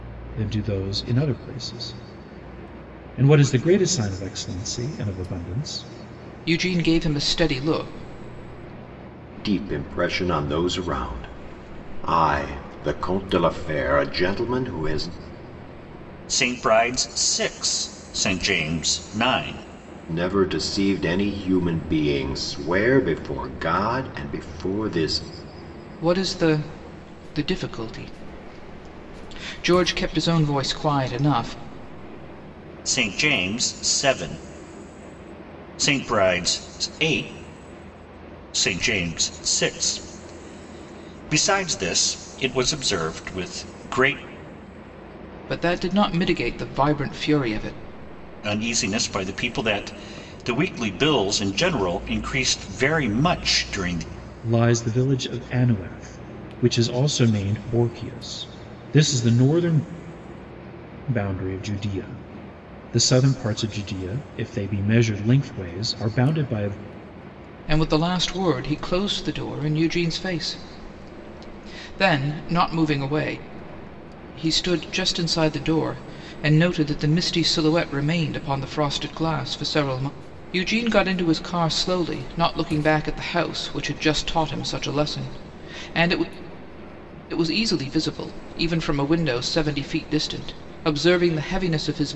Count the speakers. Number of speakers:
four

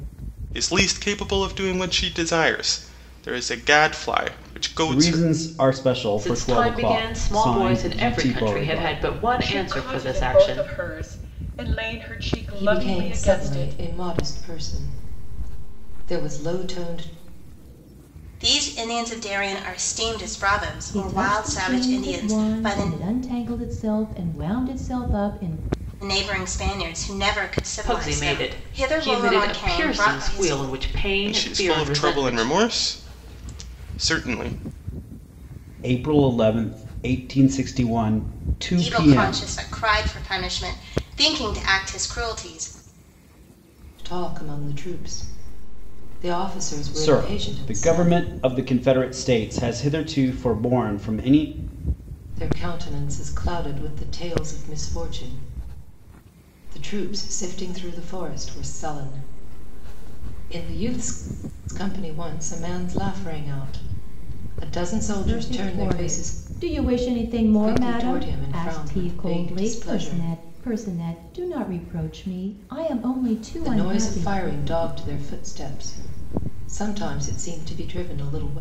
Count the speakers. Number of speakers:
seven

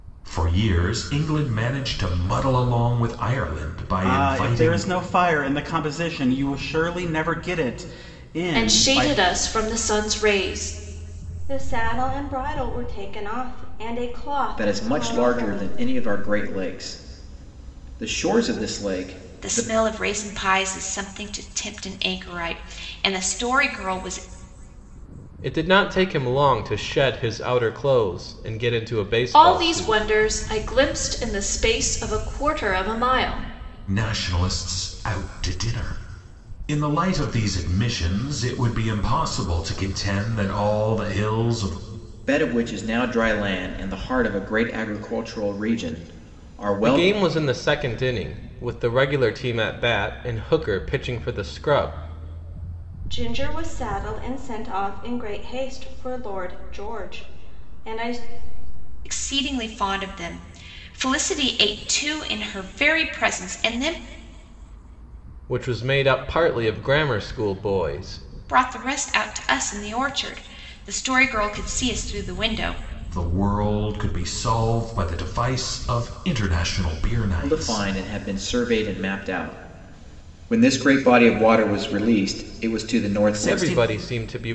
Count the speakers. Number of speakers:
seven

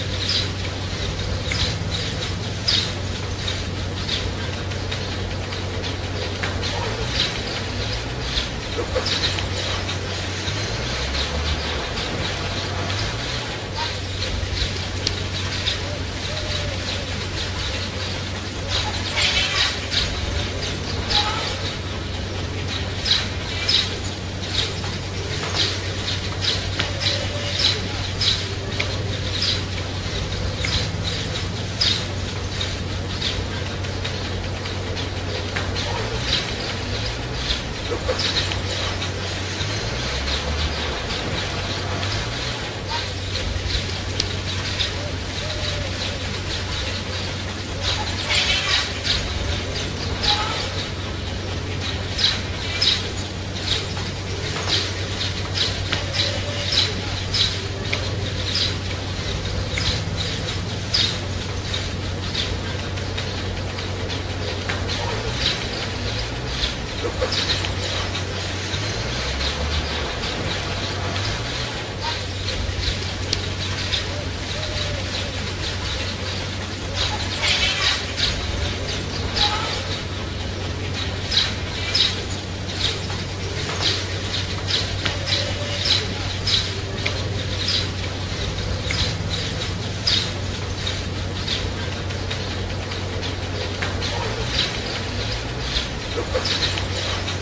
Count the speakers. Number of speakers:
zero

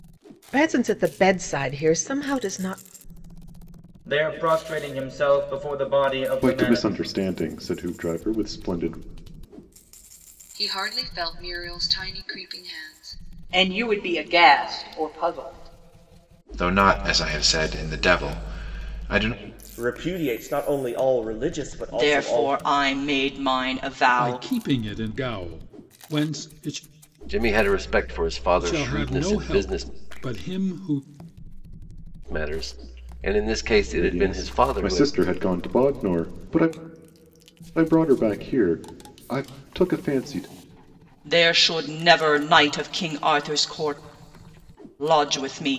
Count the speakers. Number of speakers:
ten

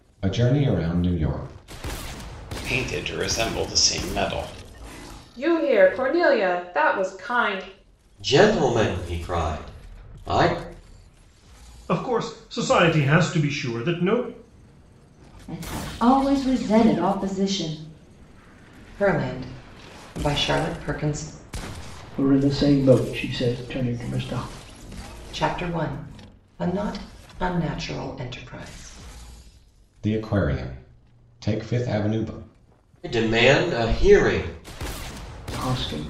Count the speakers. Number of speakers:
eight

